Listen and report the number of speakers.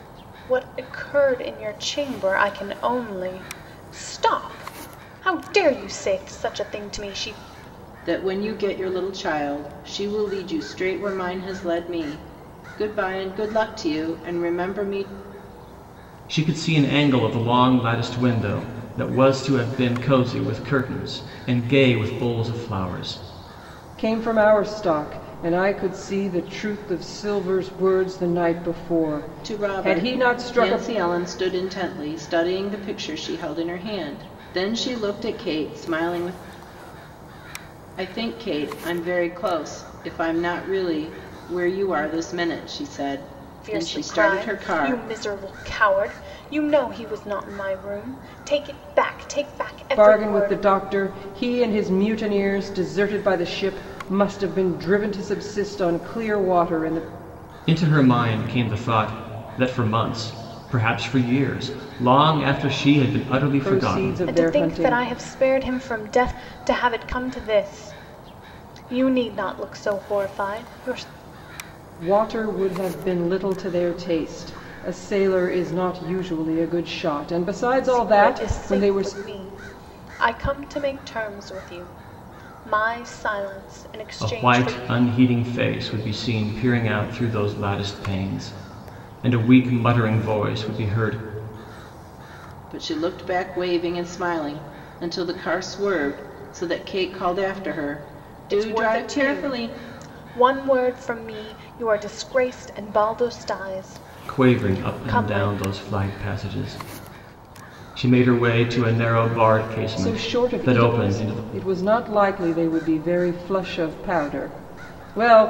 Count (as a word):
four